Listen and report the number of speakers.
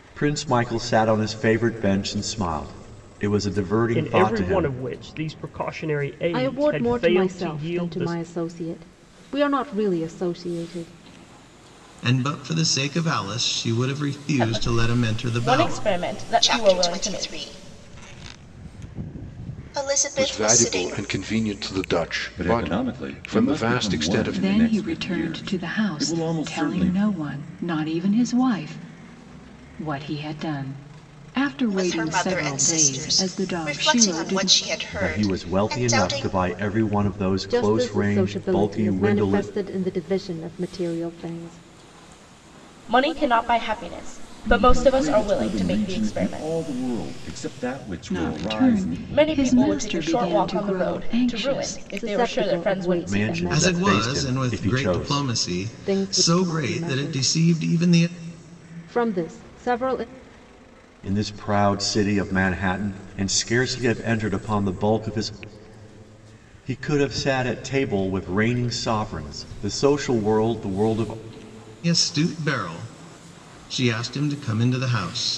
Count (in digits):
9